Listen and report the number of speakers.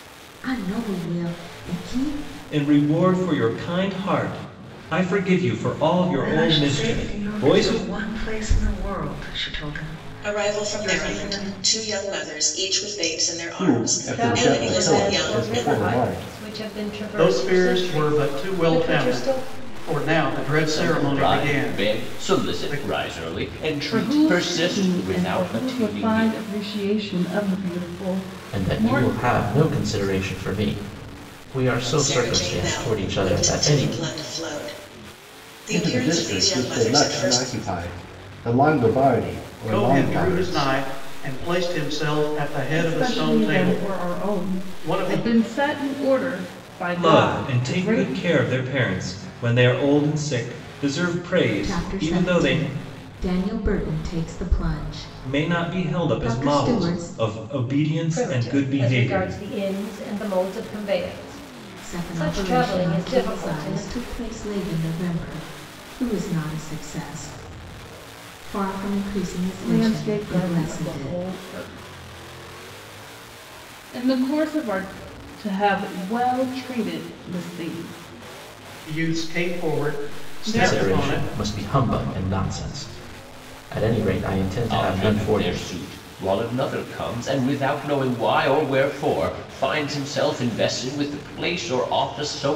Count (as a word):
ten